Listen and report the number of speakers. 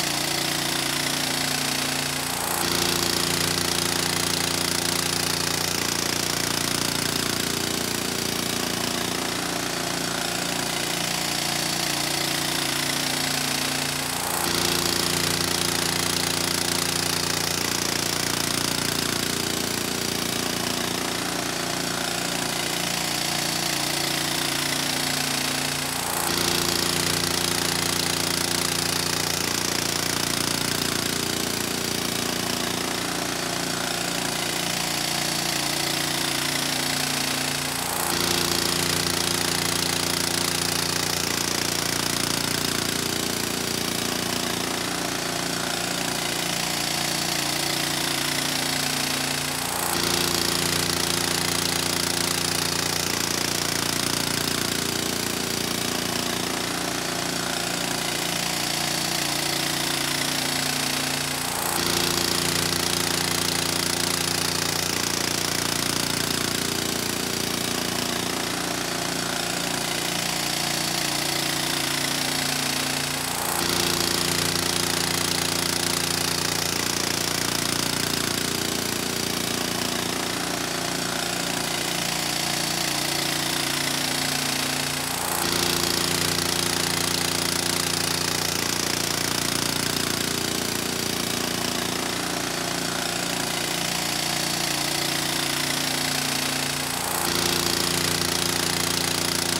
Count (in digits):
0